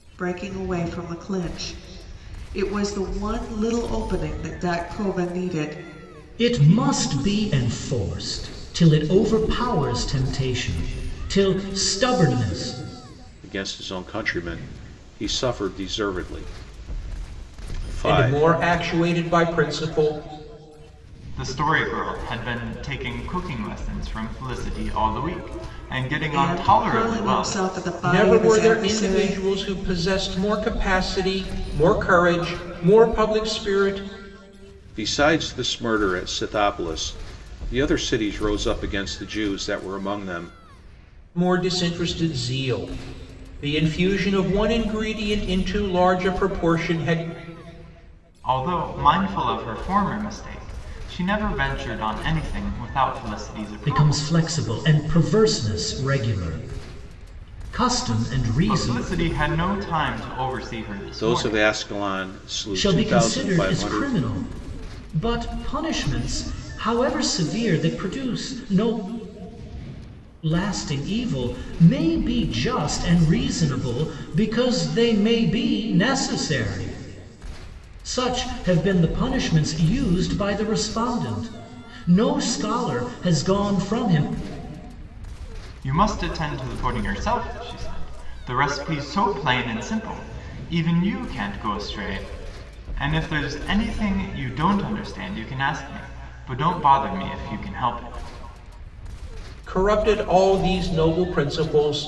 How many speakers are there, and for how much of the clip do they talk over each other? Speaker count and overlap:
five, about 6%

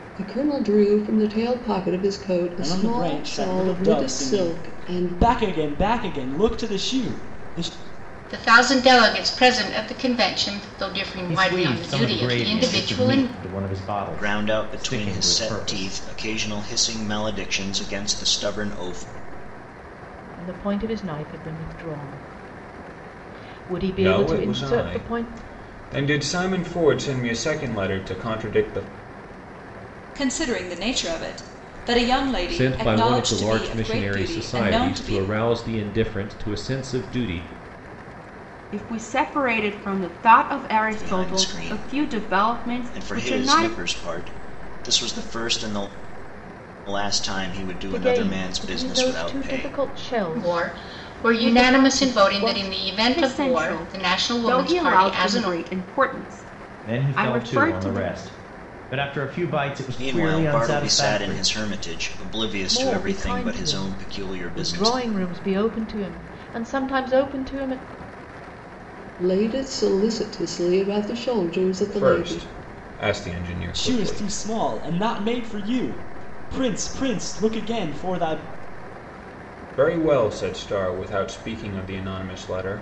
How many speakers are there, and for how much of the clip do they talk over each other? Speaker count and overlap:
ten, about 32%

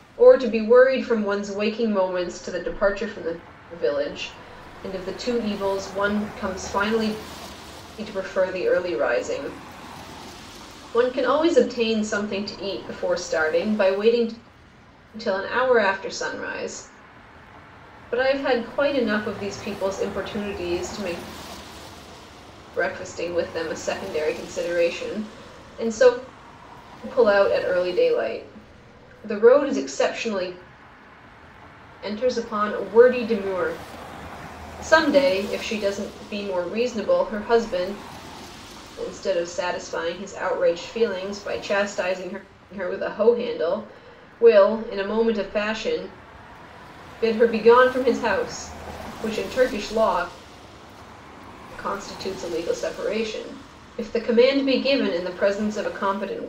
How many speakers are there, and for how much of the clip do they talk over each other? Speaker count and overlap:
one, no overlap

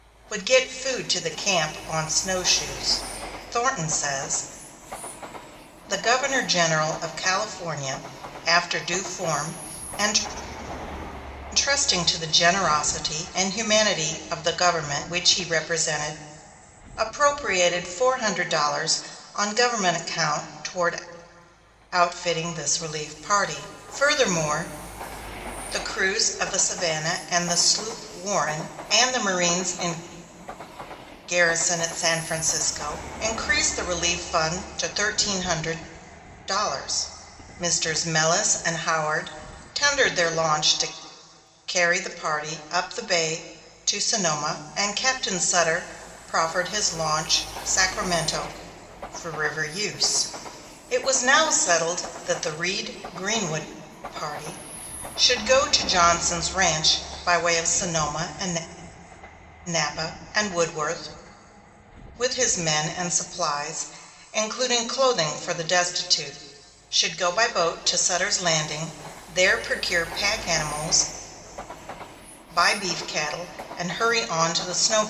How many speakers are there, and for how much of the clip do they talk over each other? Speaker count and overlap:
one, no overlap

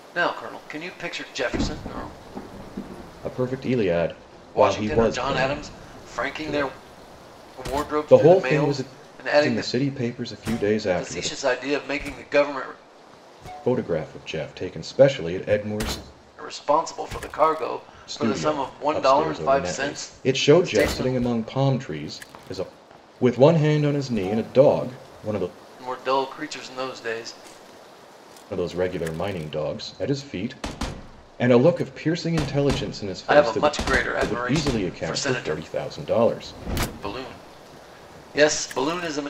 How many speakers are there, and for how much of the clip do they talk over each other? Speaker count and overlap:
two, about 22%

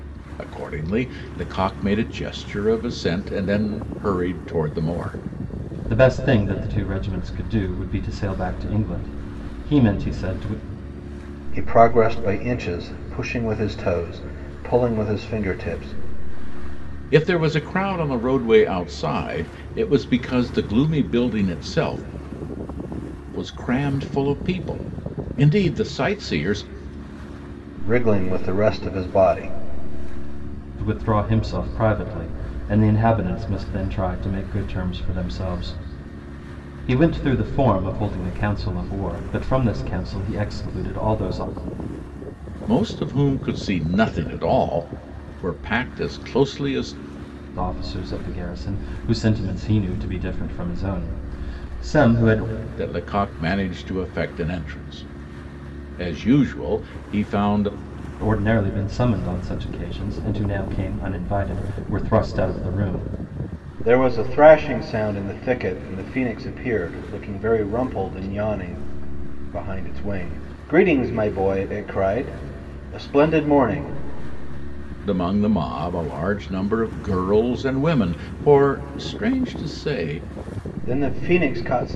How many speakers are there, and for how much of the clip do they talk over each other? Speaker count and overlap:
three, no overlap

